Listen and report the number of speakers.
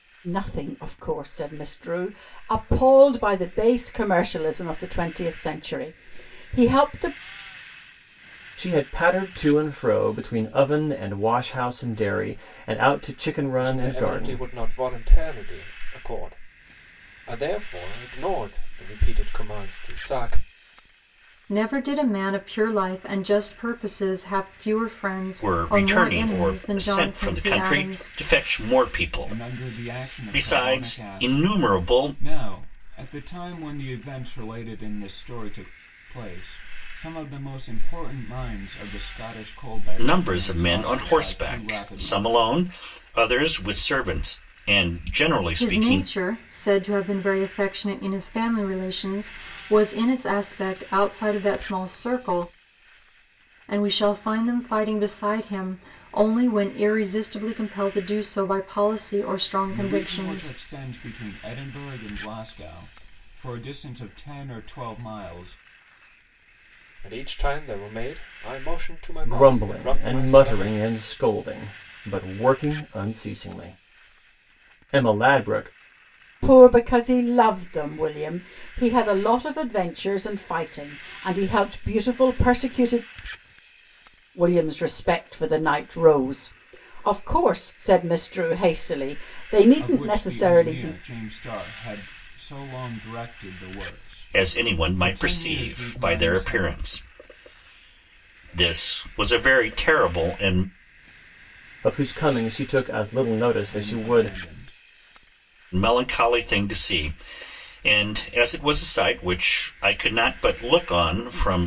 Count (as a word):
six